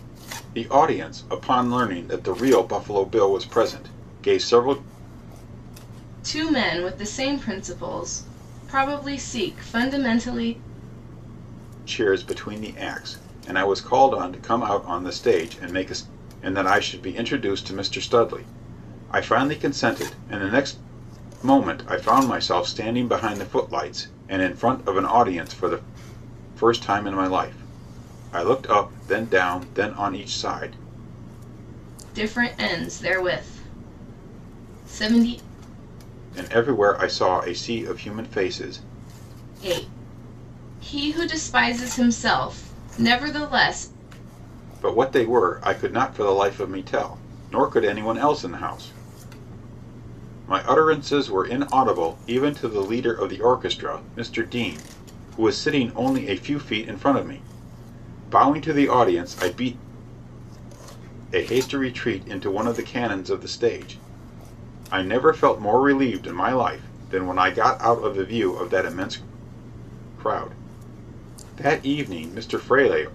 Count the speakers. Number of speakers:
2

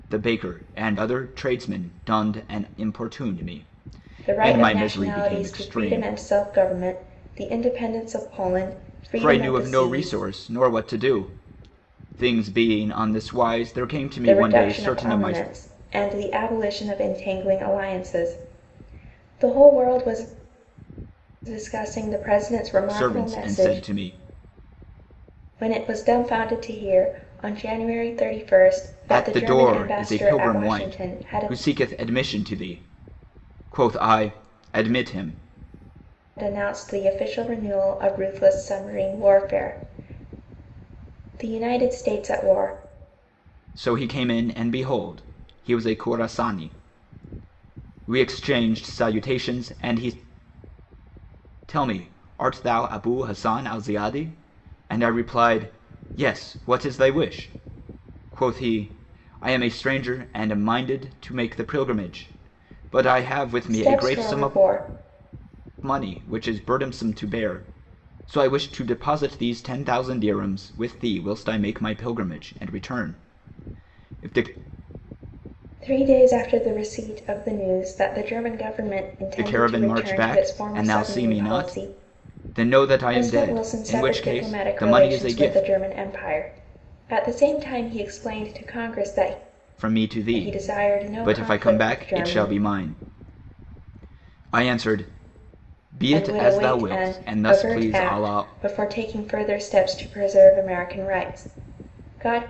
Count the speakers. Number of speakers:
2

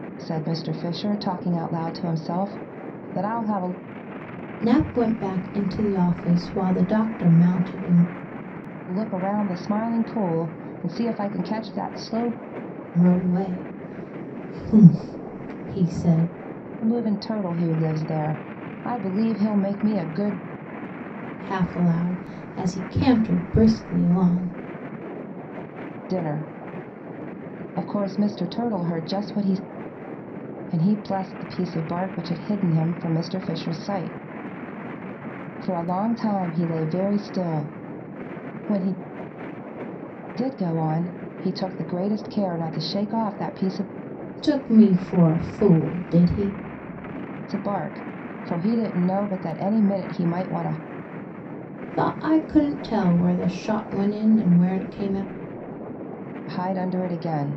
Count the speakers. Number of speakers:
2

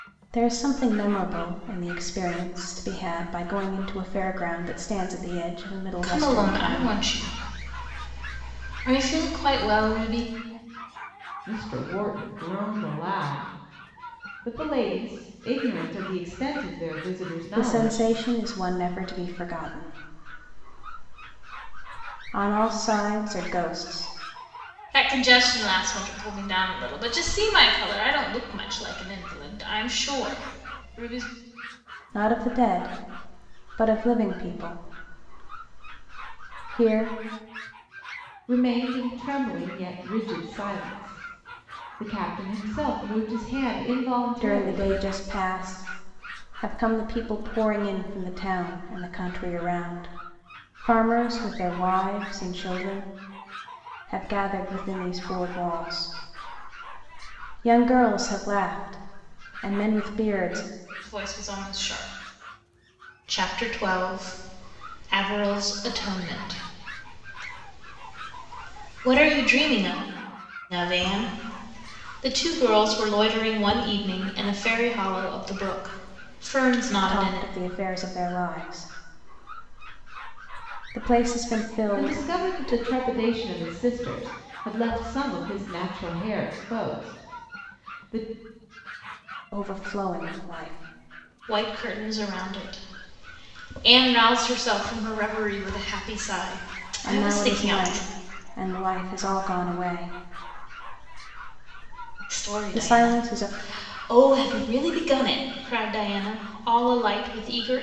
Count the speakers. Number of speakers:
3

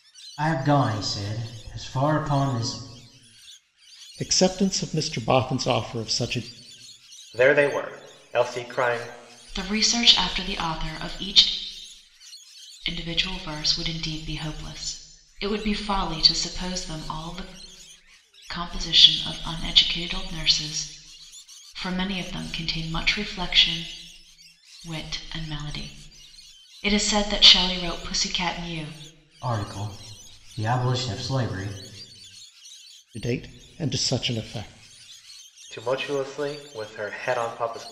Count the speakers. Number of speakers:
4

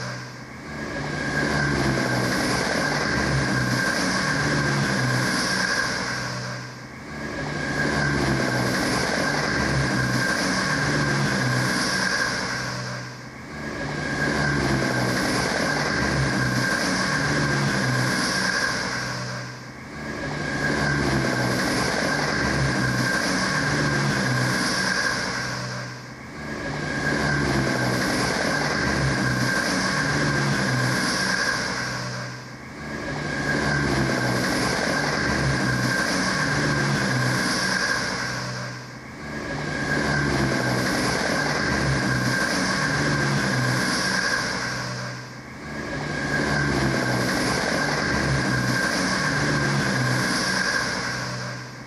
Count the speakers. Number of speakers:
0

